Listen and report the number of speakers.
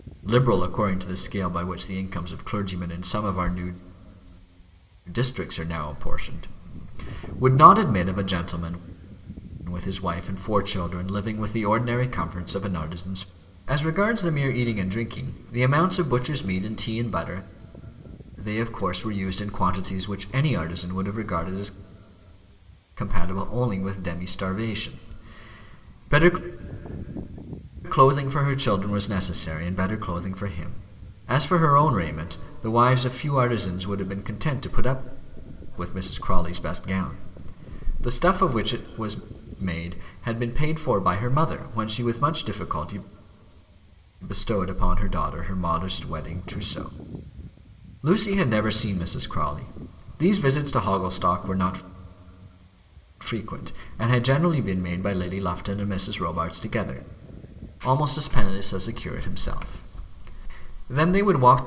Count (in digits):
1